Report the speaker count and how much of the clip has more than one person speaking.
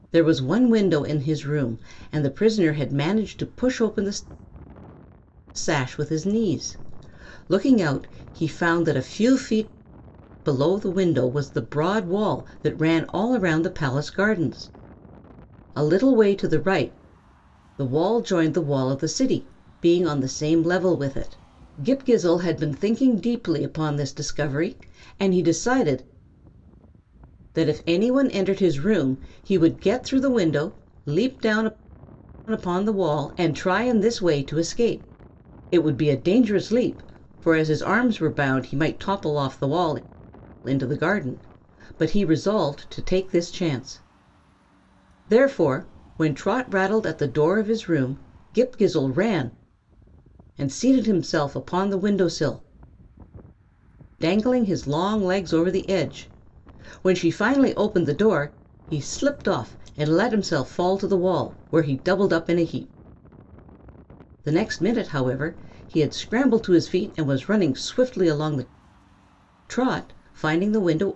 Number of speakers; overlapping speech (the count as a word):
one, no overlap